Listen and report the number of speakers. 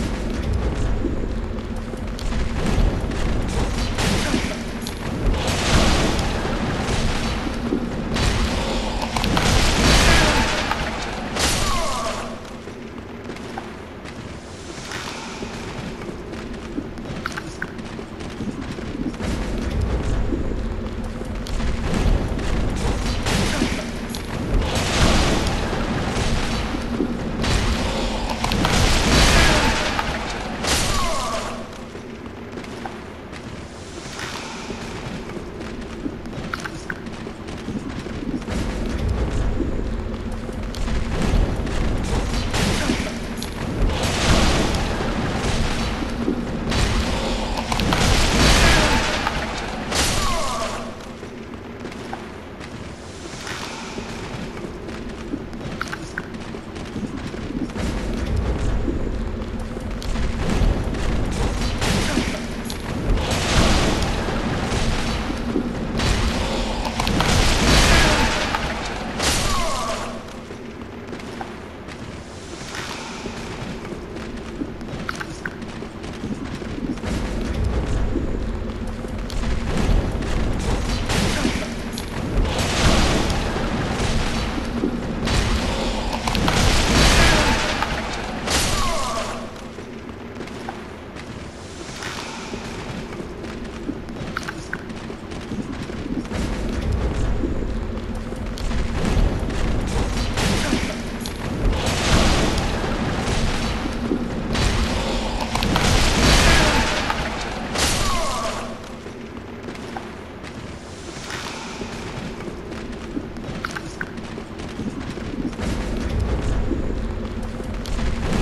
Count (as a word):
zero